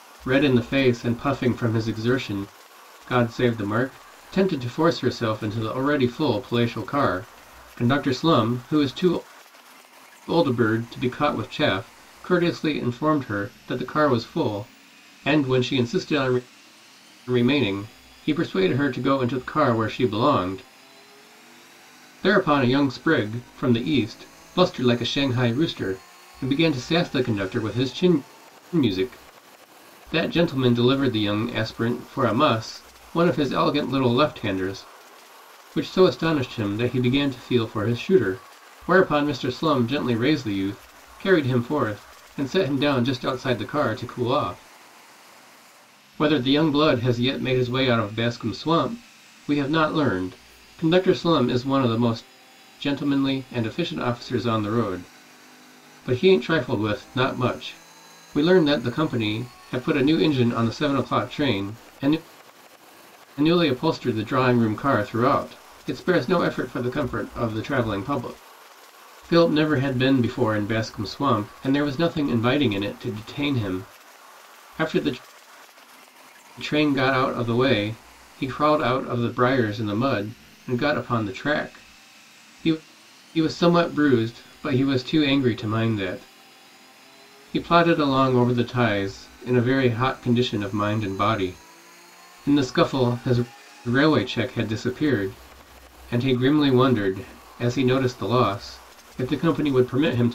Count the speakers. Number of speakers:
1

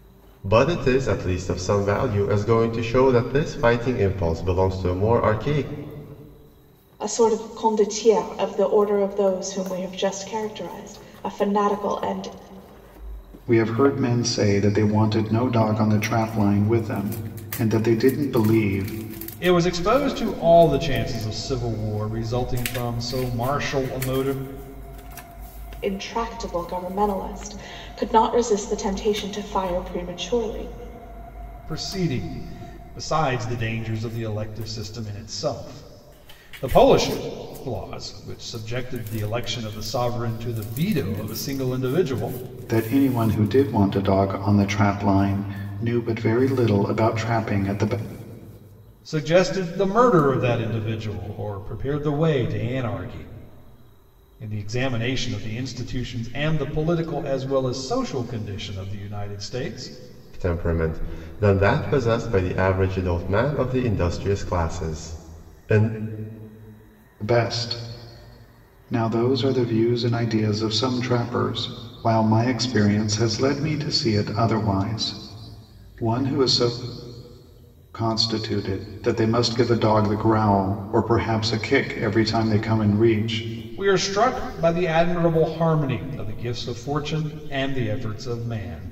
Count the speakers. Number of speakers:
4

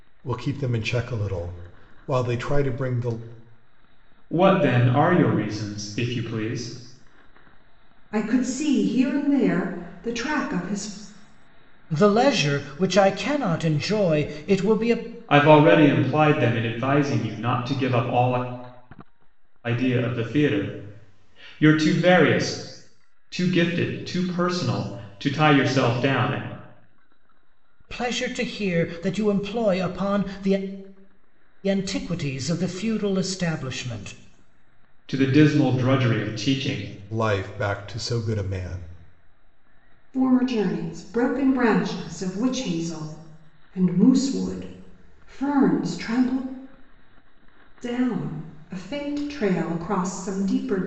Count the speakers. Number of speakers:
4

